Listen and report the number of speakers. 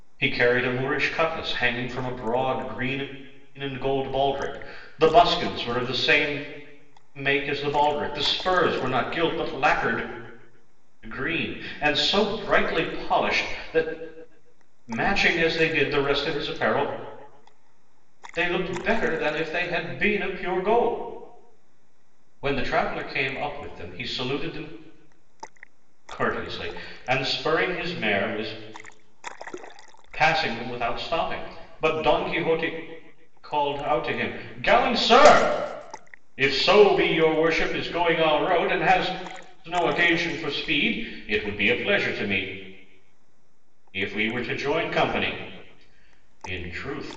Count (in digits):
1